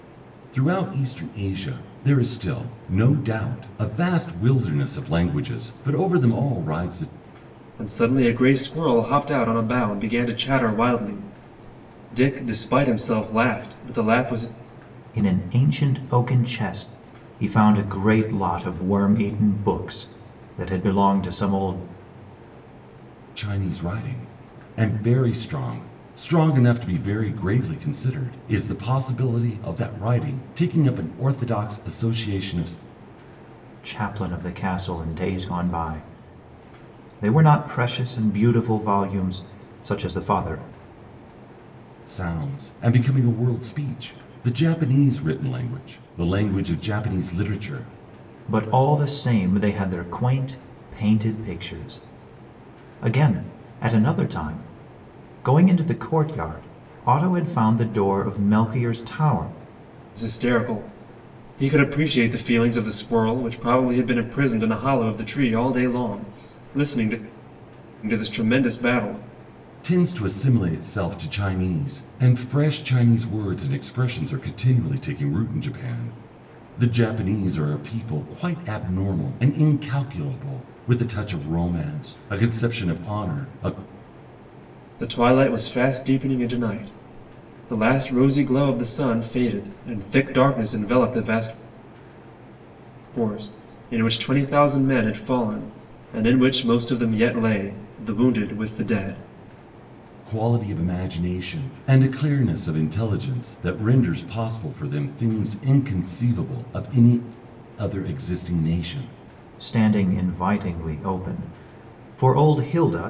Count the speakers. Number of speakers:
3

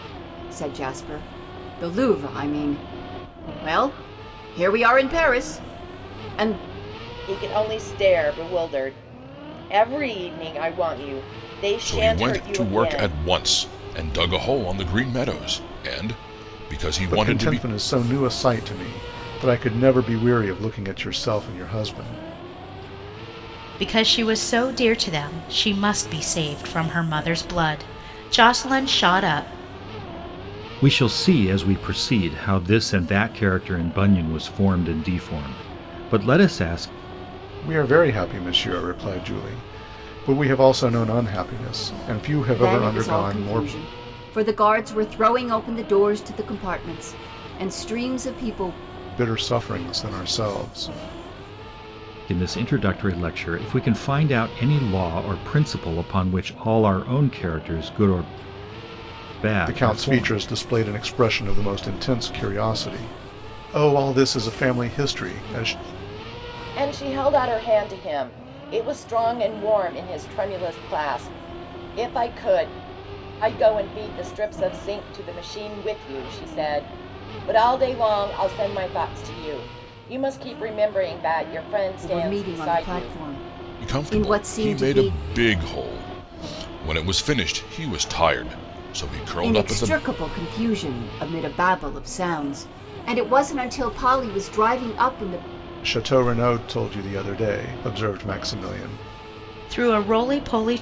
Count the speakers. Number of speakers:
6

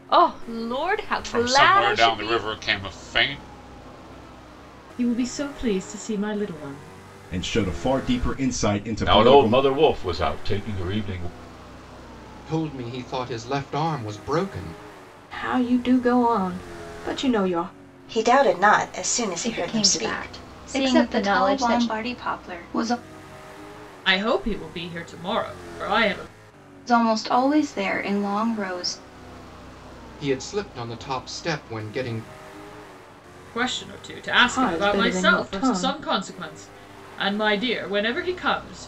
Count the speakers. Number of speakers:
10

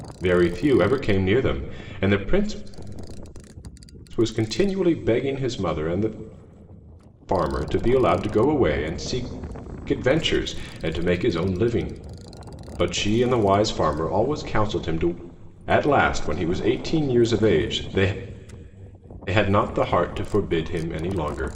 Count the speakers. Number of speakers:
1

